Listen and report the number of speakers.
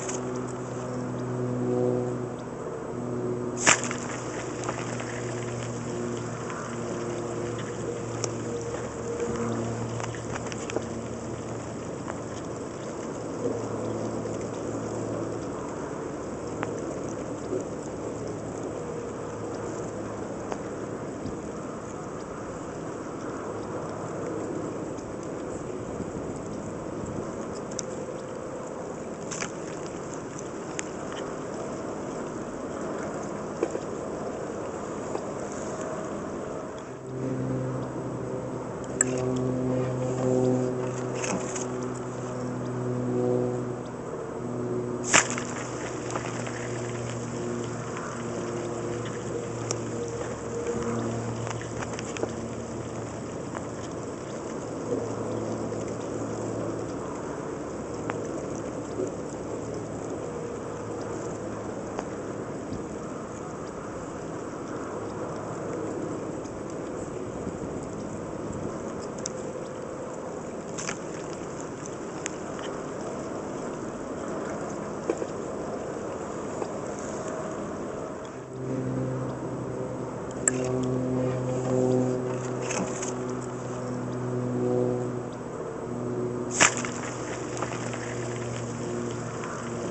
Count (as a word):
zero